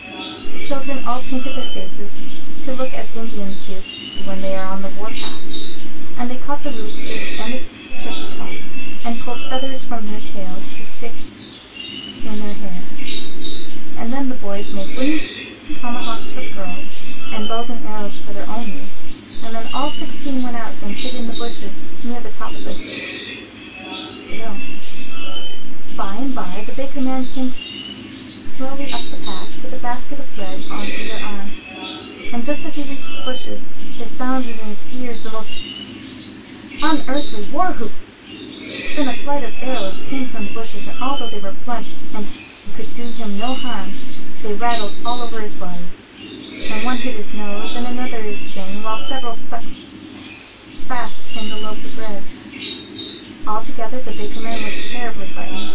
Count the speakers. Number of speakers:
1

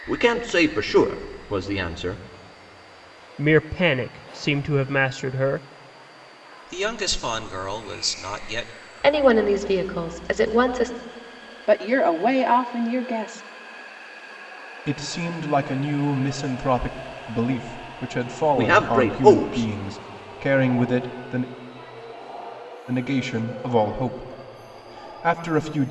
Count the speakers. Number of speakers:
6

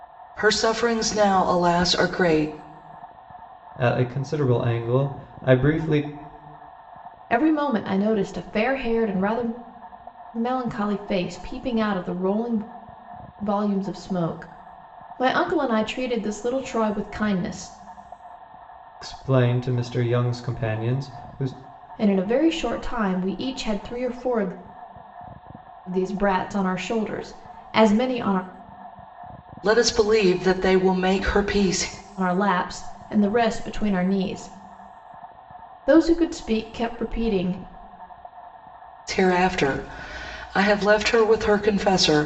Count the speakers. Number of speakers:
3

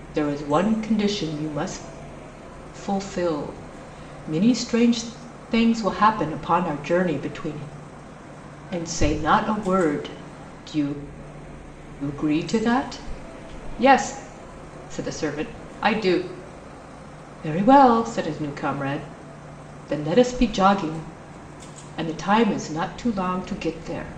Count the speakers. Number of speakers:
1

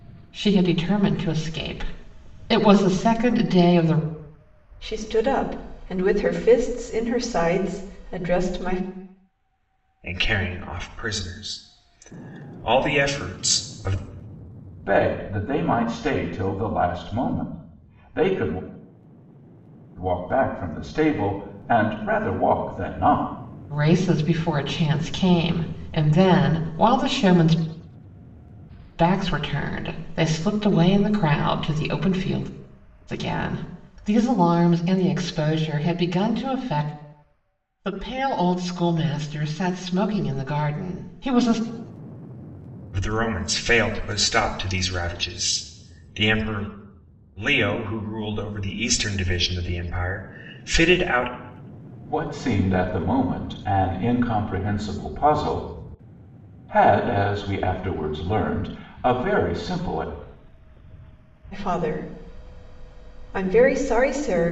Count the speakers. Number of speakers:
4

